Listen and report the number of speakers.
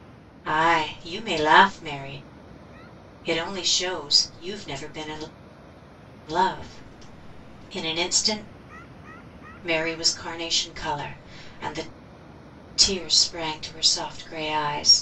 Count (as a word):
one